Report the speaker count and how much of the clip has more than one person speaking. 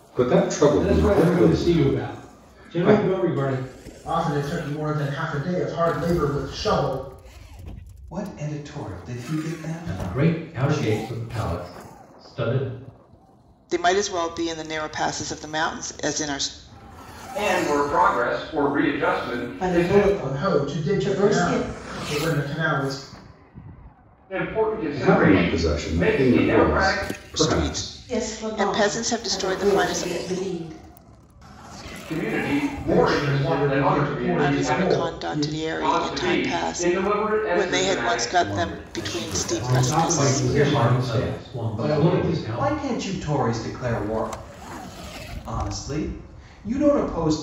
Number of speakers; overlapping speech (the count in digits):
8, about 41%